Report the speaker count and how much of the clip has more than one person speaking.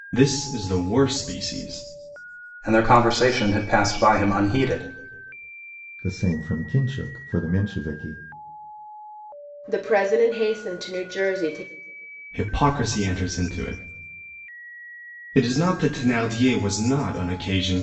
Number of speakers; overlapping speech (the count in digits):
4, no overlap